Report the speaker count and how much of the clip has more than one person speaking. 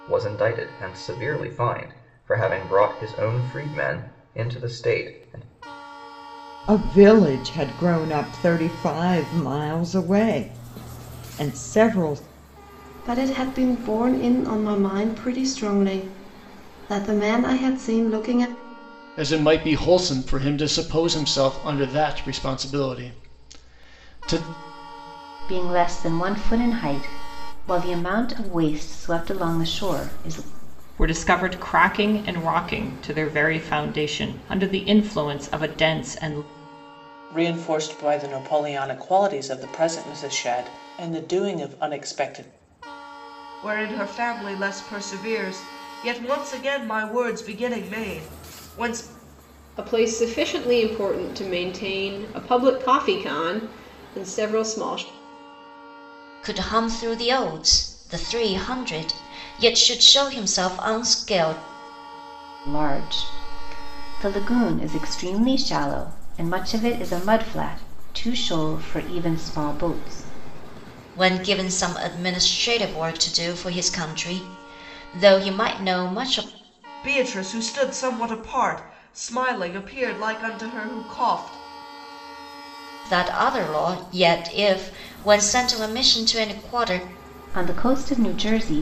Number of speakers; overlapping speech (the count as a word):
ten, no overlap